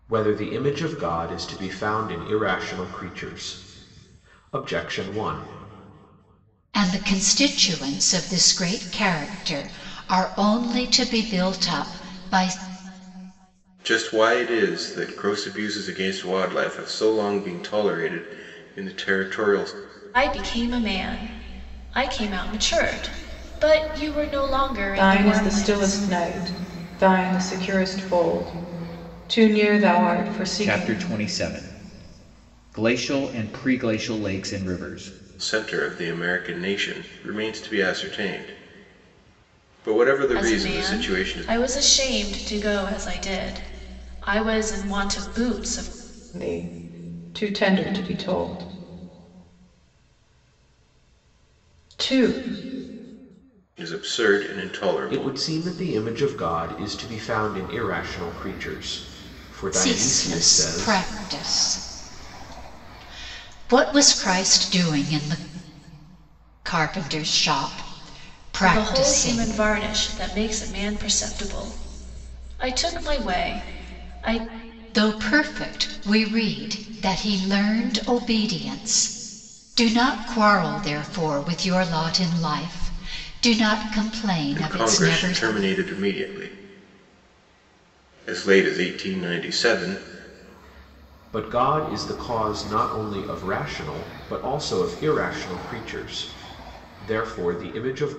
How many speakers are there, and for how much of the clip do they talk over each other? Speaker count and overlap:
6, about 6%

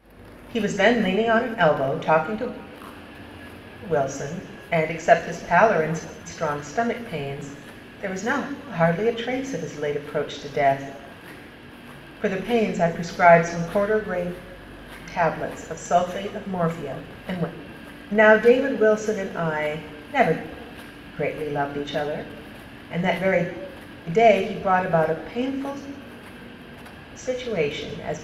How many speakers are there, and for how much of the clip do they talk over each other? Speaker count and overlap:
1, no overlap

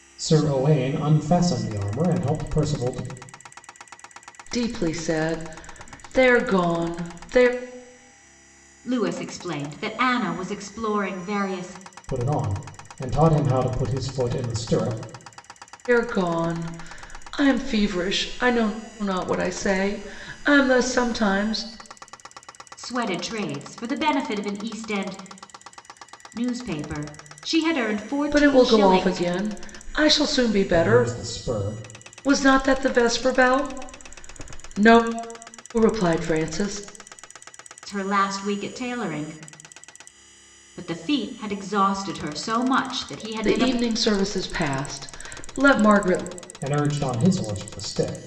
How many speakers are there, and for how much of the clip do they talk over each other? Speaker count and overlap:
3, about 4%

